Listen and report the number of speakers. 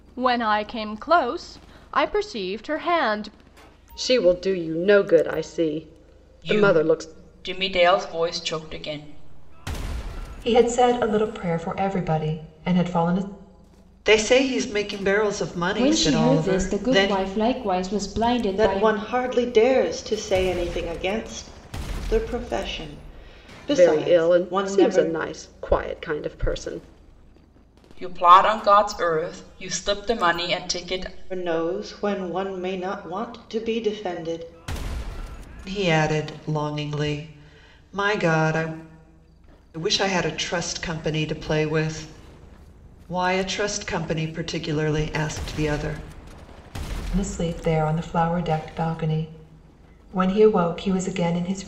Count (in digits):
7